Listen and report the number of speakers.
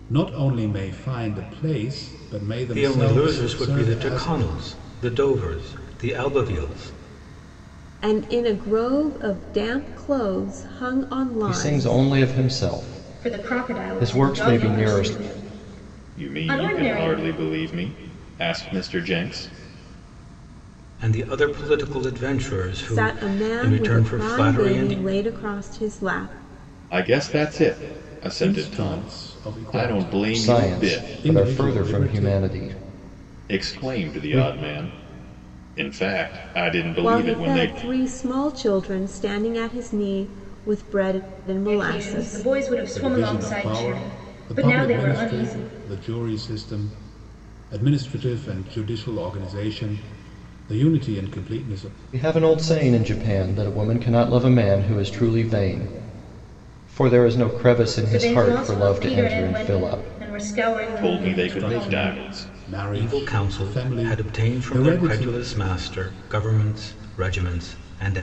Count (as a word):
six